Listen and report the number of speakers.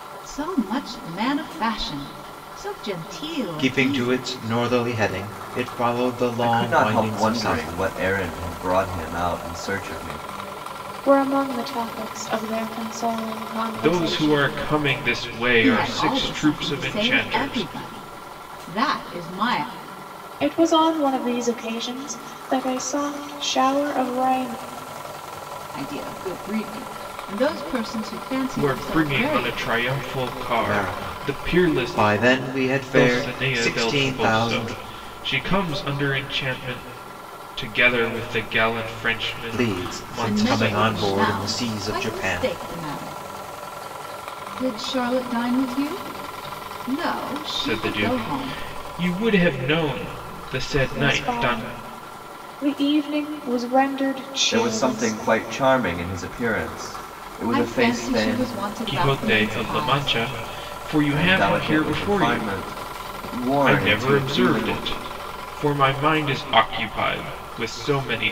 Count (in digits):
5